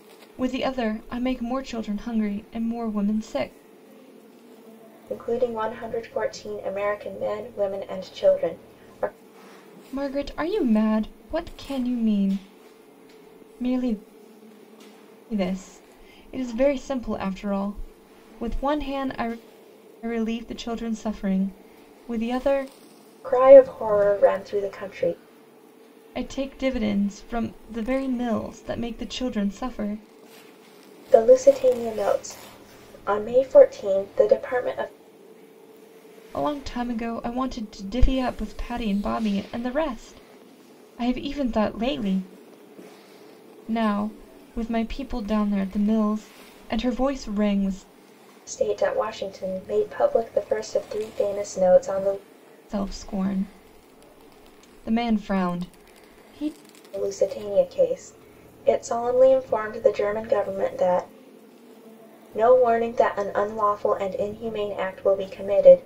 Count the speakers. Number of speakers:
2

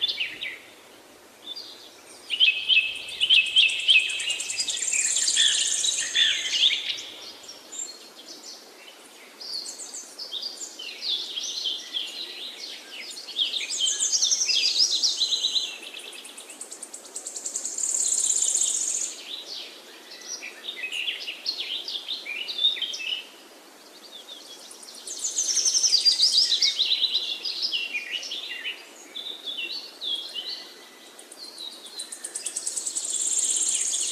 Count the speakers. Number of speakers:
0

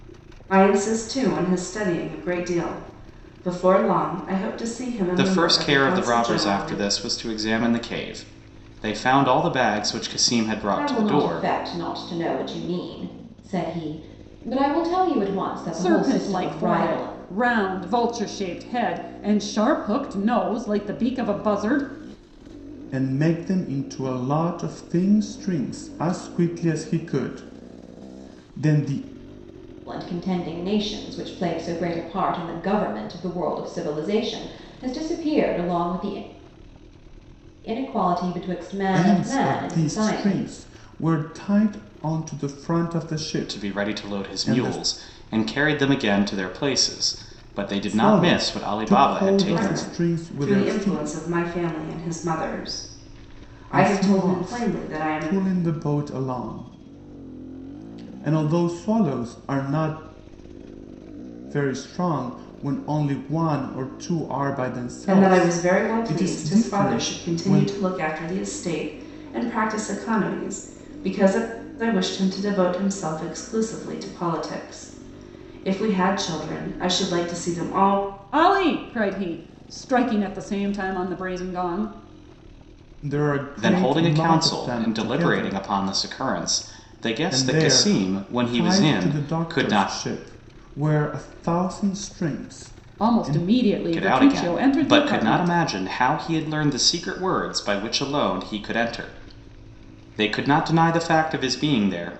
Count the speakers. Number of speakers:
5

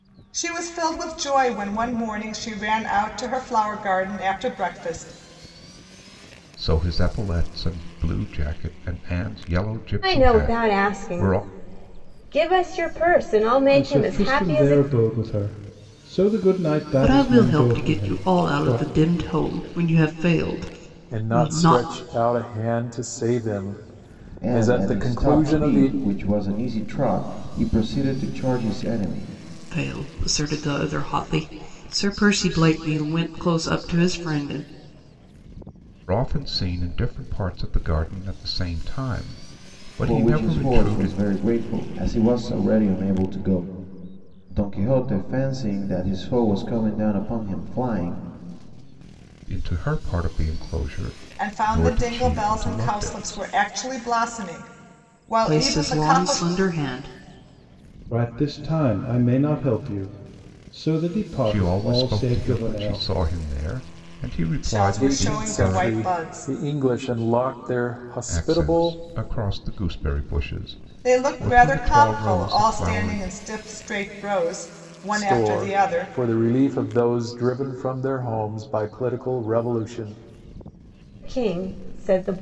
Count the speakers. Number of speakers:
7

